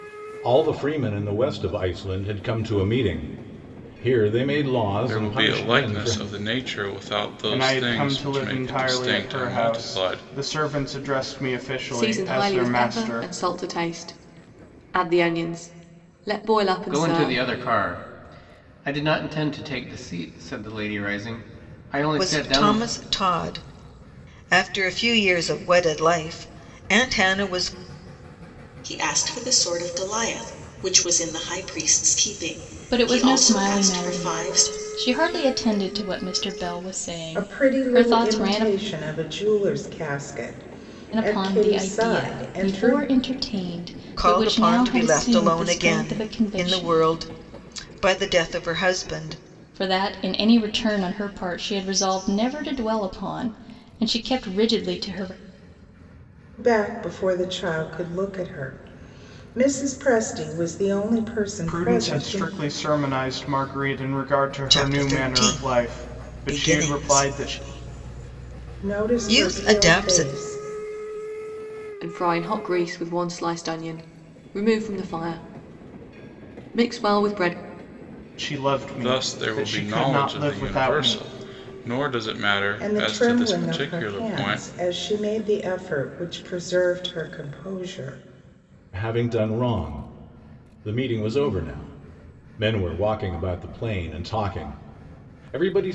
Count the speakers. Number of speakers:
9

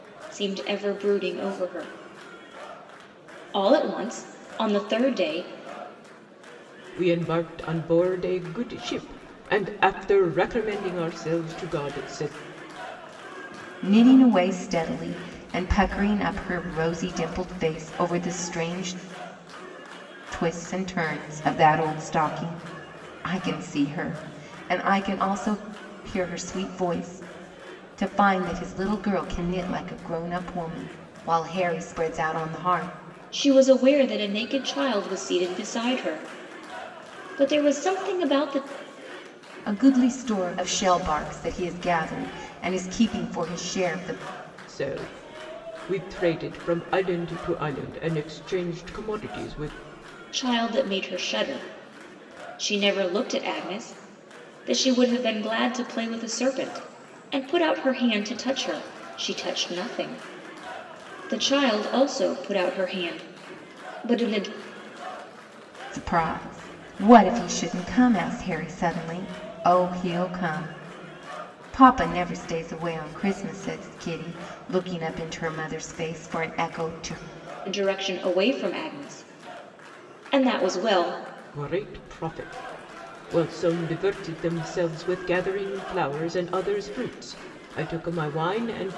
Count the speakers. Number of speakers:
3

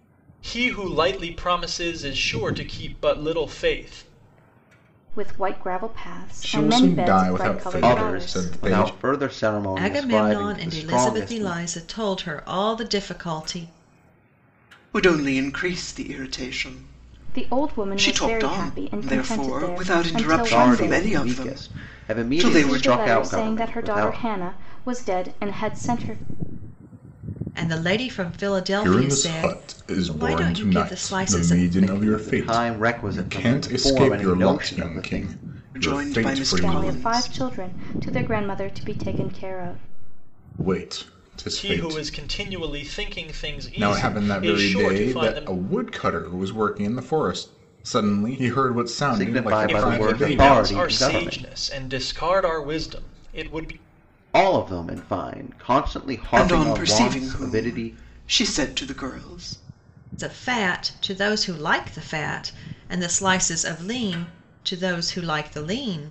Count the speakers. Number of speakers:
6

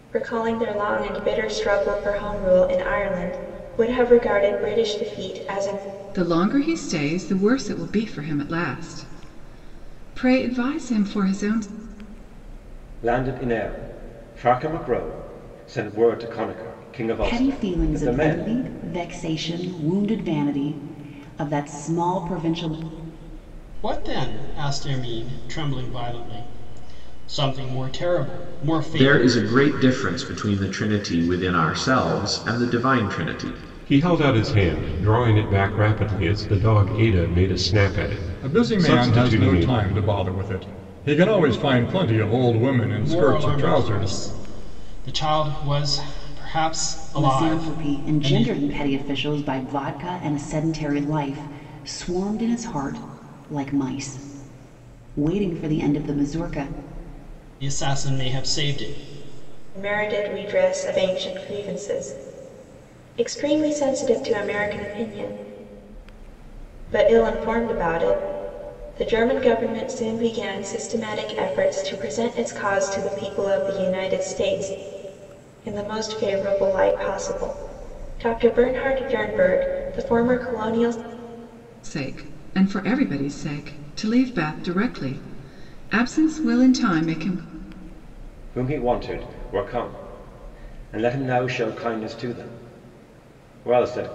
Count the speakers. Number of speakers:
8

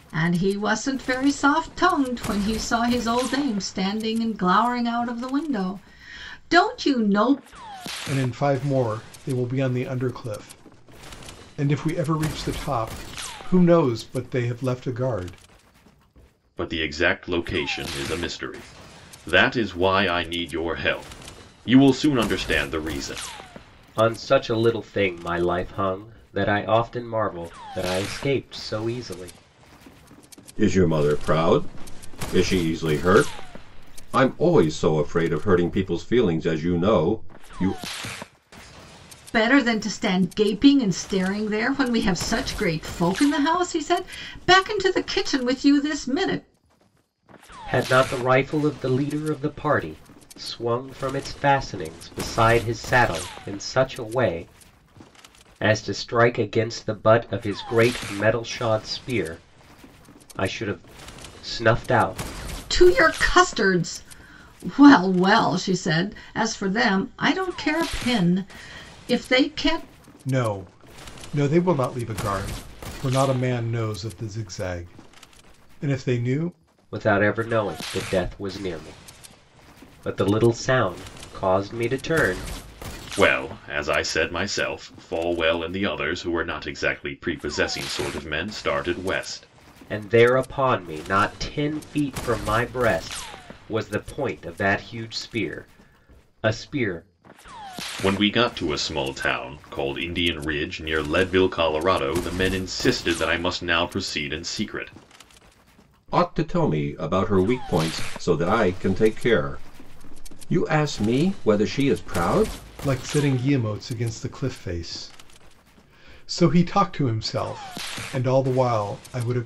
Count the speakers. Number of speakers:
5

